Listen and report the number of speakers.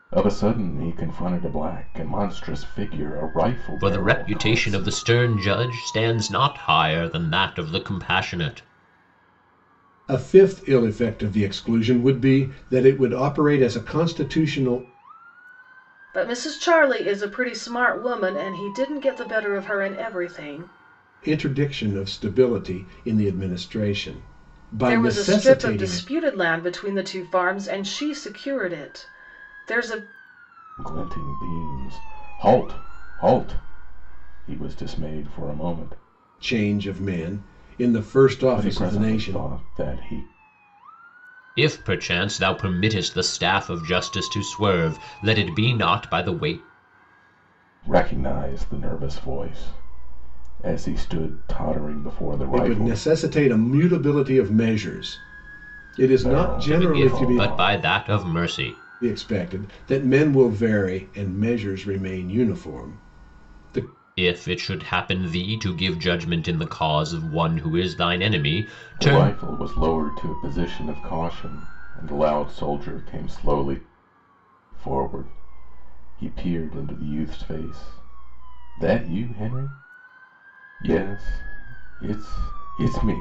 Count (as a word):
four